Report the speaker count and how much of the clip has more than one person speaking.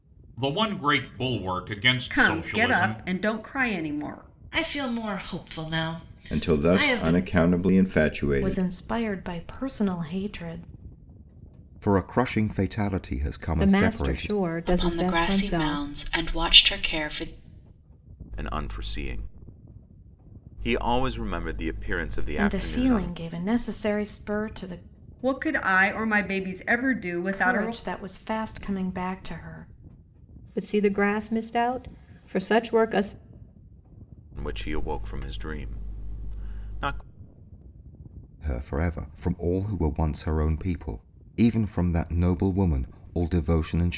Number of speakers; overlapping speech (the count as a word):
nine, about 13%